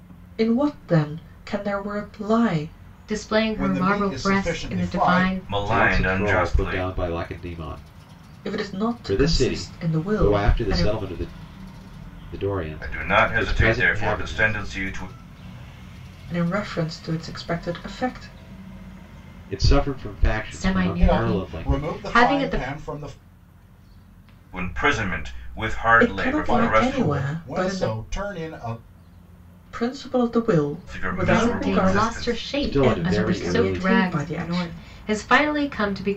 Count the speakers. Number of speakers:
5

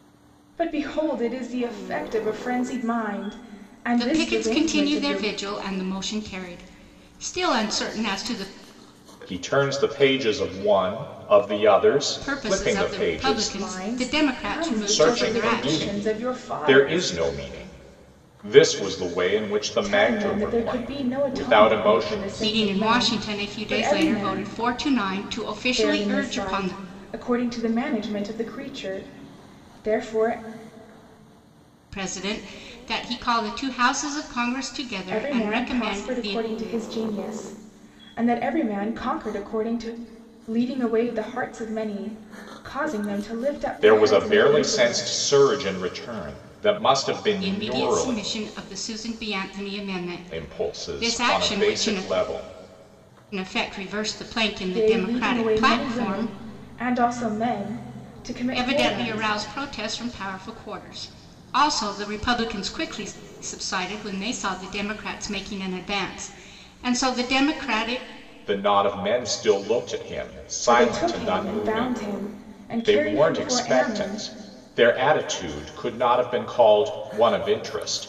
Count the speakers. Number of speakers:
3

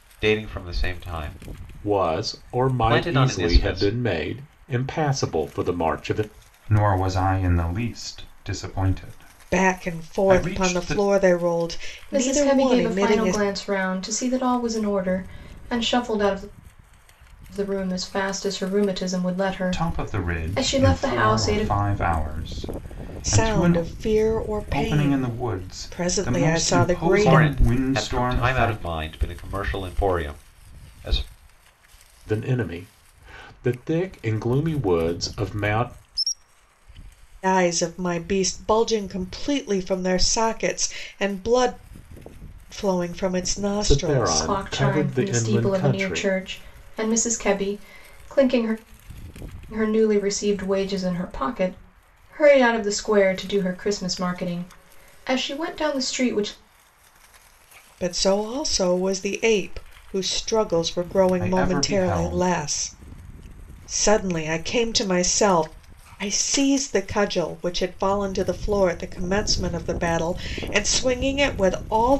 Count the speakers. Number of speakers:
5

